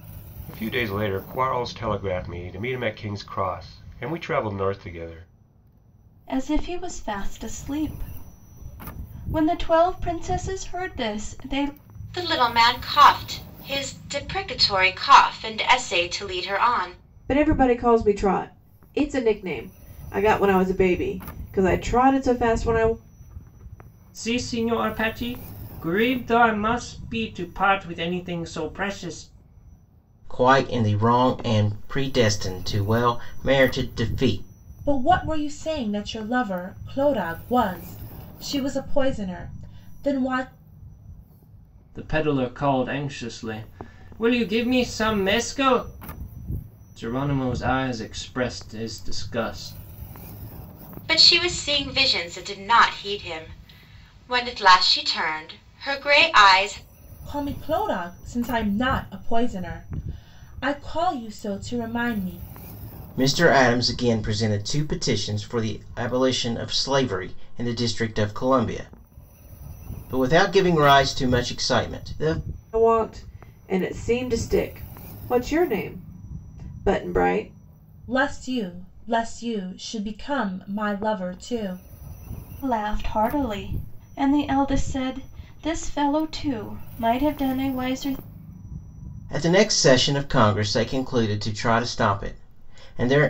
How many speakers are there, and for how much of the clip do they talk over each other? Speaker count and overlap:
seven, no overlap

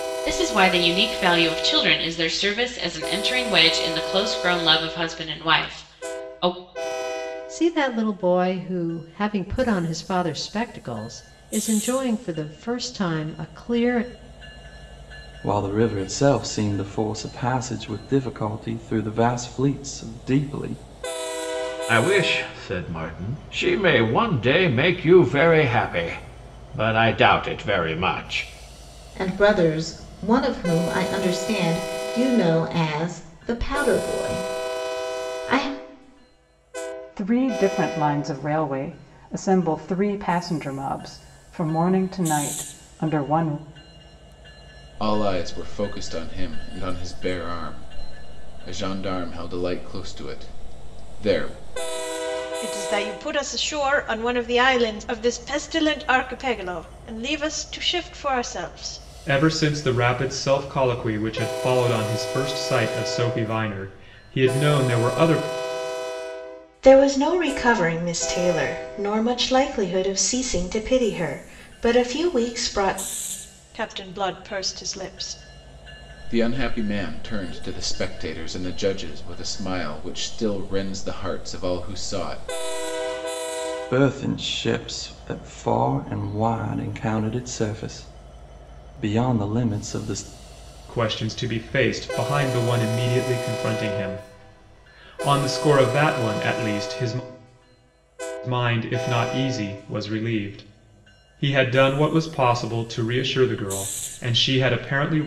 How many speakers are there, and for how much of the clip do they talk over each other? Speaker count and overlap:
ten, no overlap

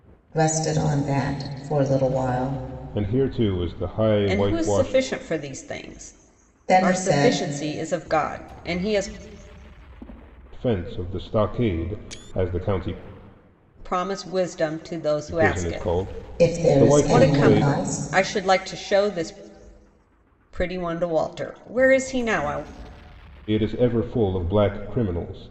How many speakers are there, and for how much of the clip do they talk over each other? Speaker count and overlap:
three, about 15%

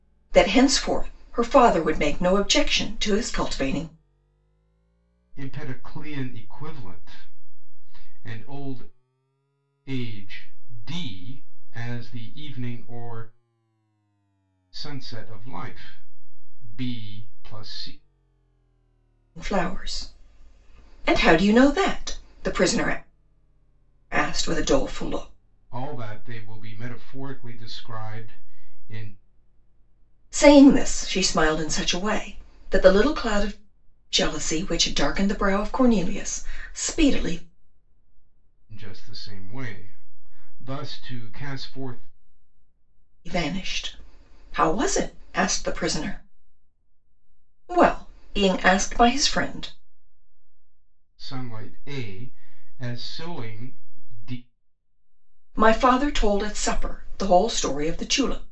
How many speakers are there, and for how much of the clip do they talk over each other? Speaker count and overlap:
two, no overlap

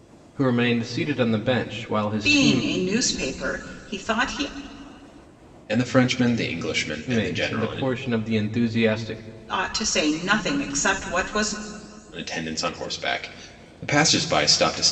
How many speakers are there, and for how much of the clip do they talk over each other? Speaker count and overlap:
three, about 9%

